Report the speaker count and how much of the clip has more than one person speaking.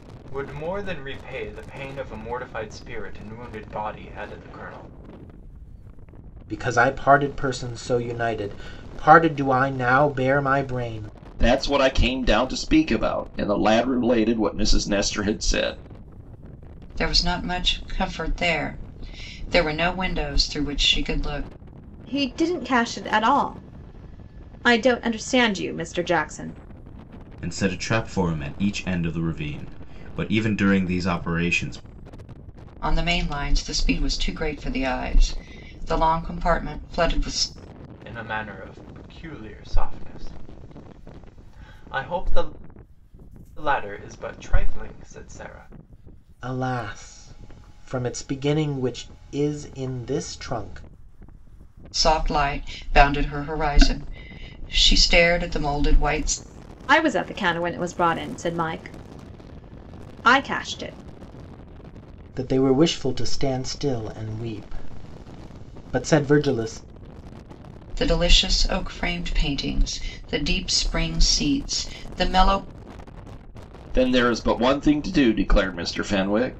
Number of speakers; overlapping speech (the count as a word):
six, no overlap